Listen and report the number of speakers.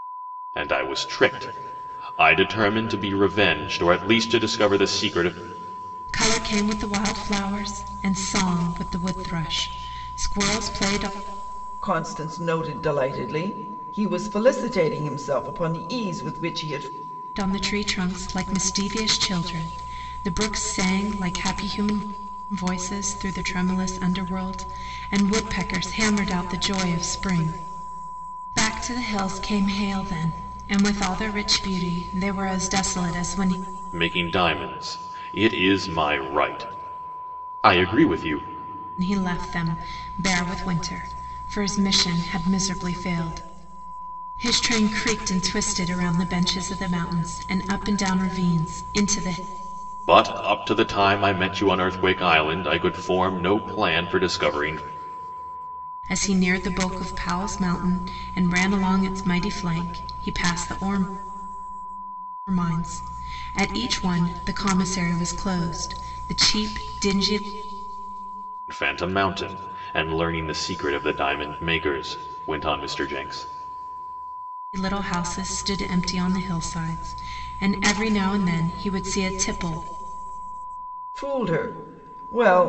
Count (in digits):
3